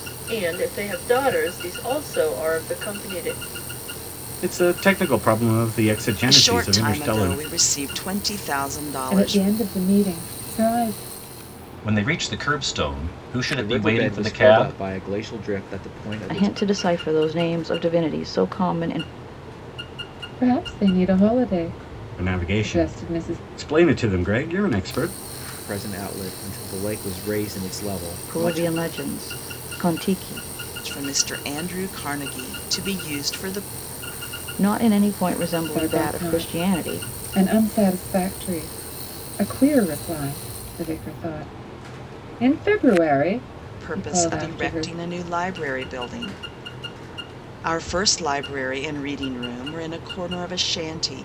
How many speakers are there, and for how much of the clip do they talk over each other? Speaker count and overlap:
7, about 14%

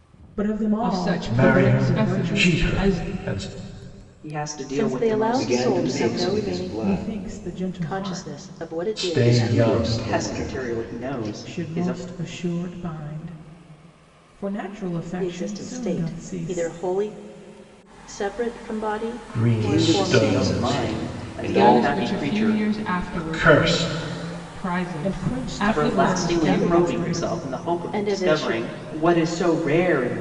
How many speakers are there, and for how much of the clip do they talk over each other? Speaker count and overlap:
6, about 58%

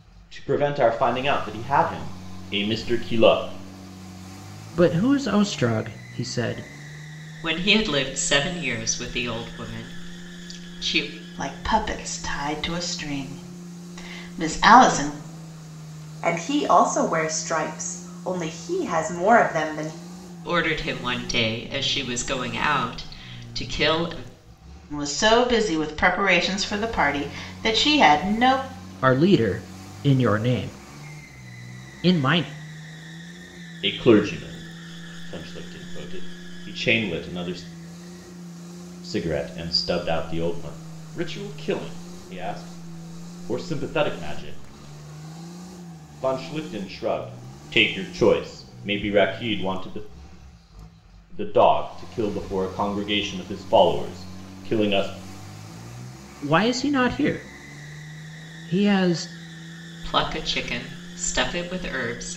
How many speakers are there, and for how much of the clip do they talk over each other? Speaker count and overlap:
5, no overlap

